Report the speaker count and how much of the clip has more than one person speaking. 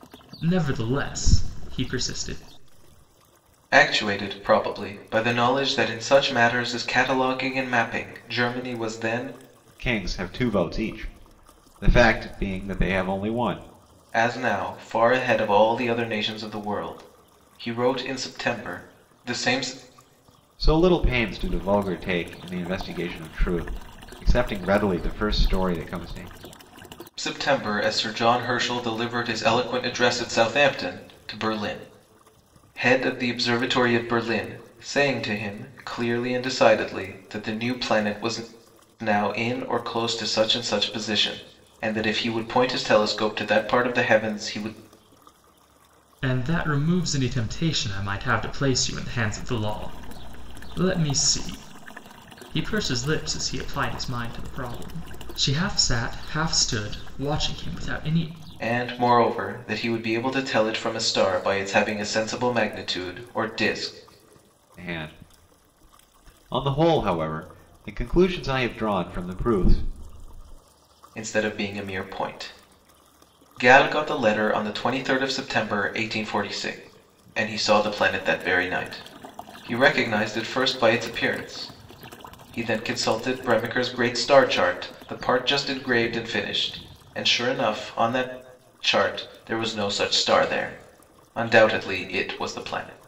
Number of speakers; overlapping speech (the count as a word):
three, no overlap